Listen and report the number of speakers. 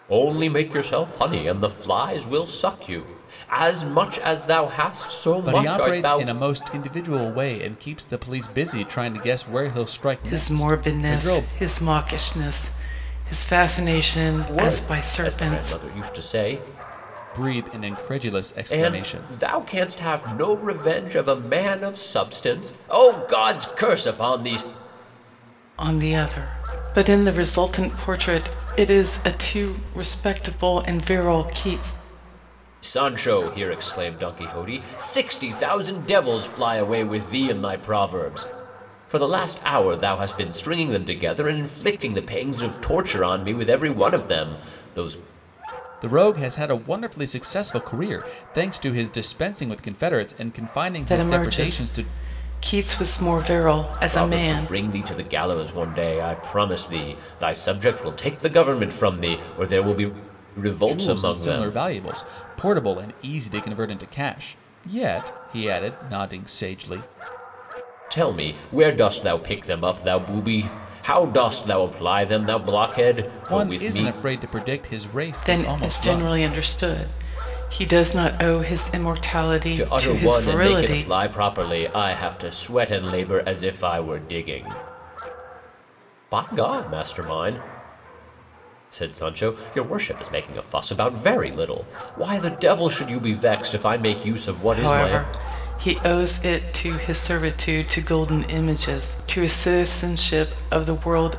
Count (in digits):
3